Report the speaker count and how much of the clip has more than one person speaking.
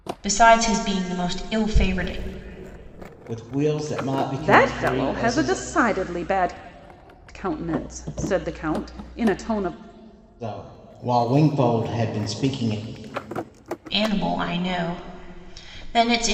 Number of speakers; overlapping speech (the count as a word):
three, about 7%